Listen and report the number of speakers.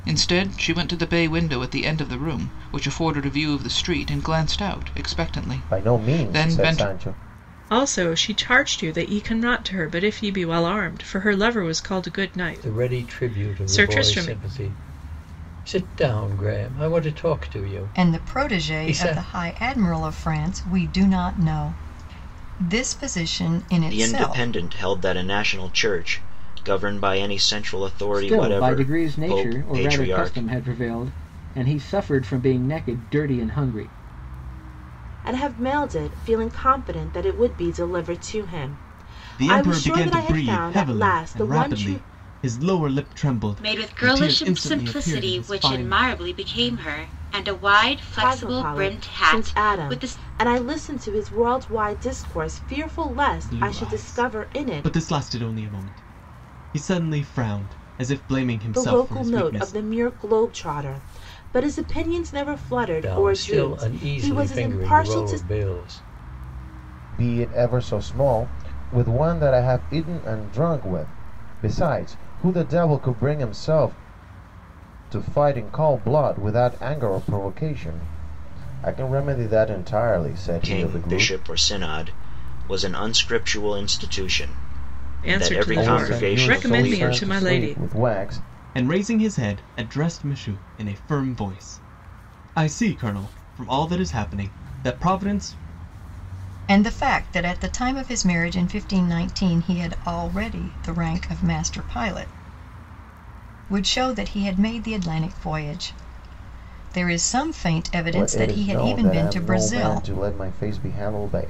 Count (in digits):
10